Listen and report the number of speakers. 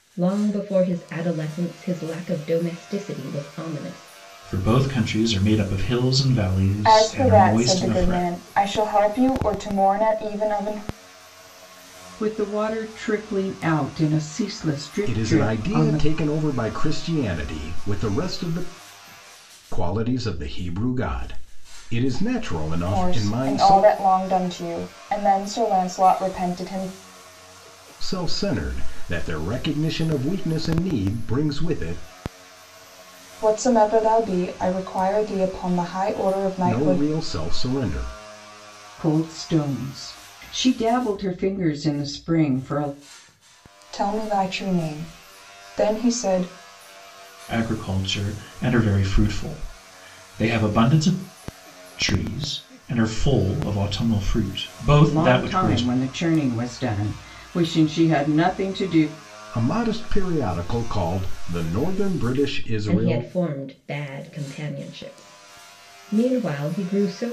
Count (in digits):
5